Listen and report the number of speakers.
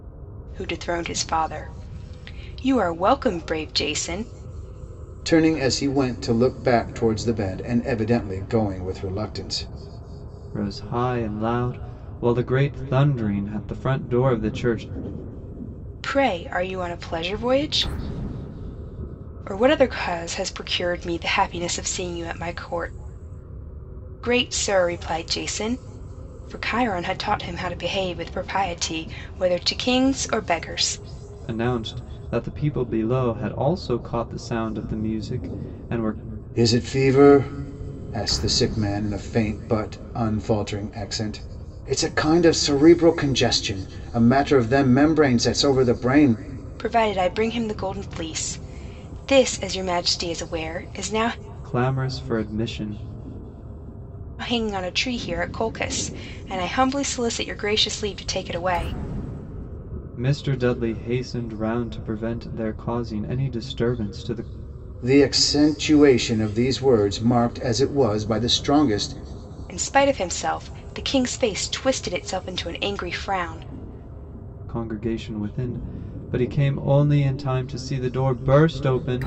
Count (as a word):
three